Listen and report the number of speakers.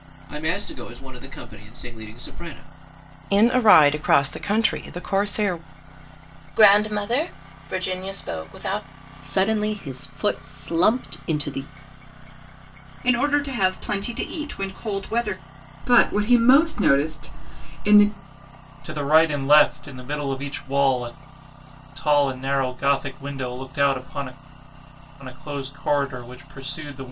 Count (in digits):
7